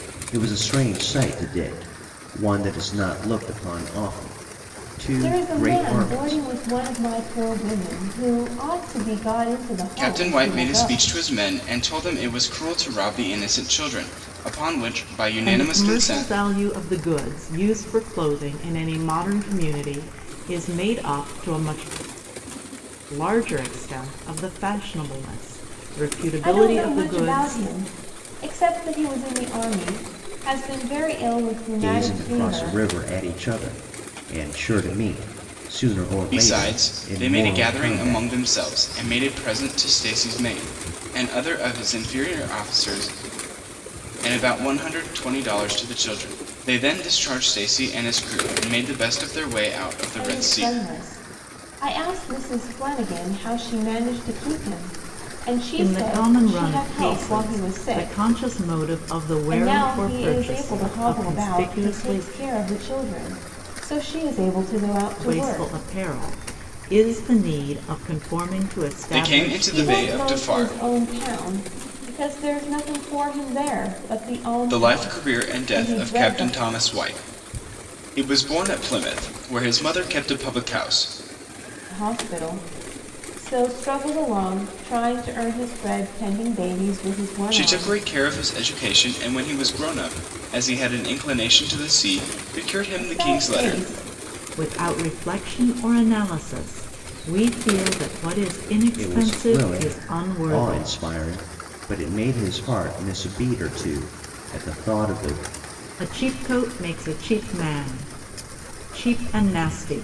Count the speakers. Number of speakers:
4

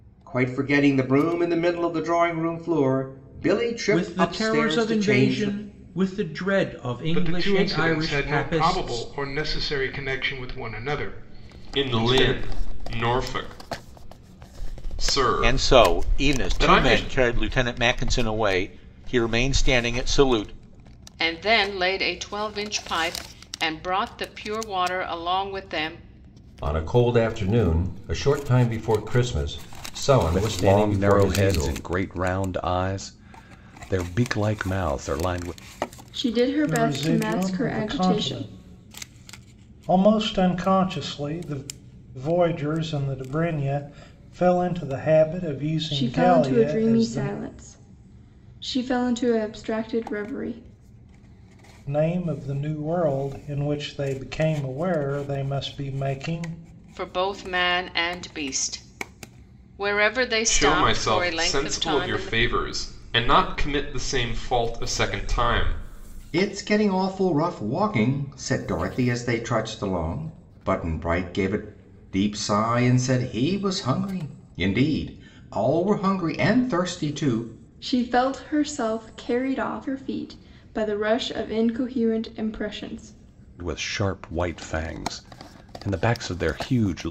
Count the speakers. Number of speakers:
10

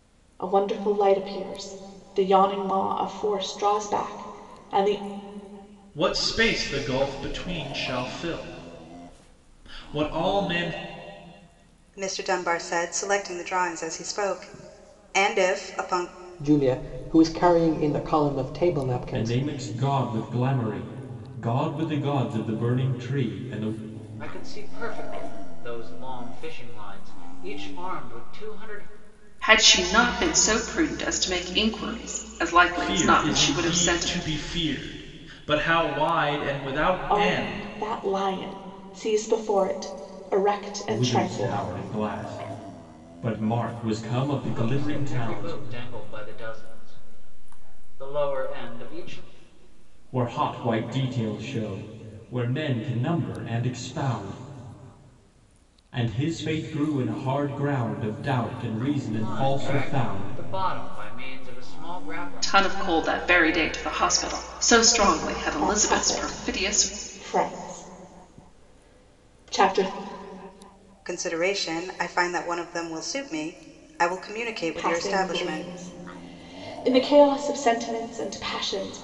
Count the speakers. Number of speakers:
7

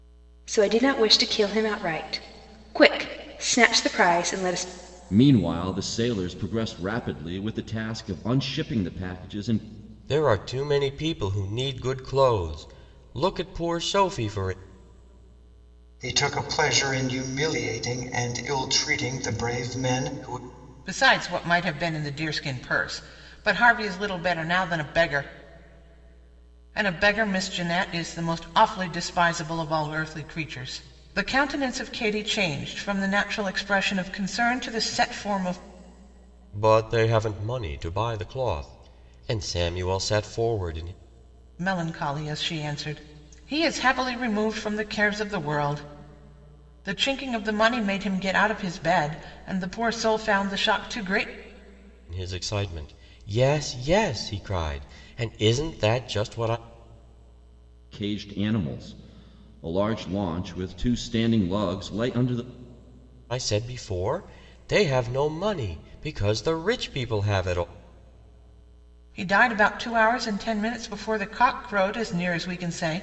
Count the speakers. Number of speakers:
5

